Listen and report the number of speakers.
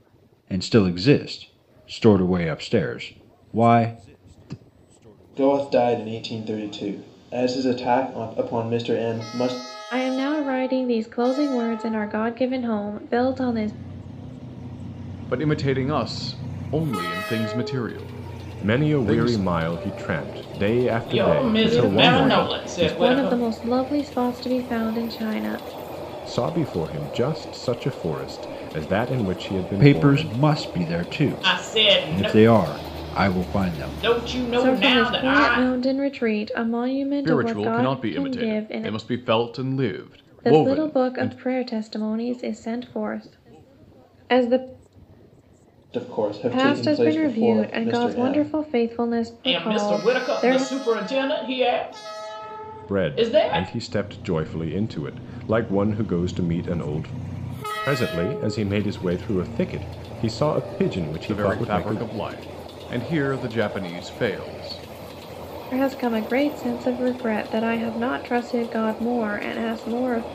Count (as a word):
six